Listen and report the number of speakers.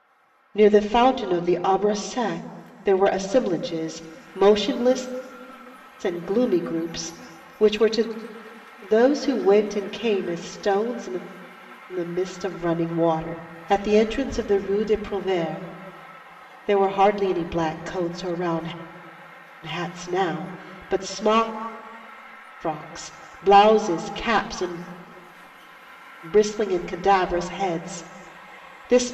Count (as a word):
one